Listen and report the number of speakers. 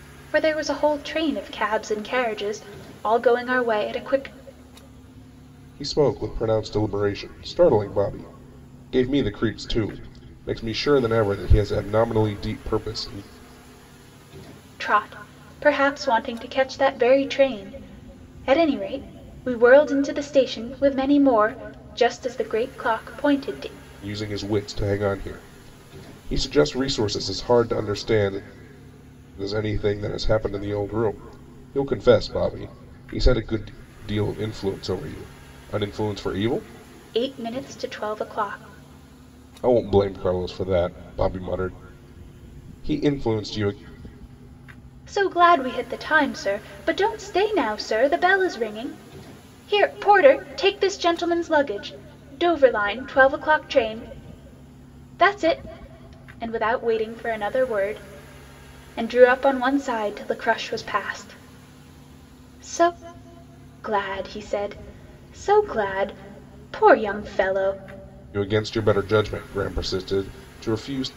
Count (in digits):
2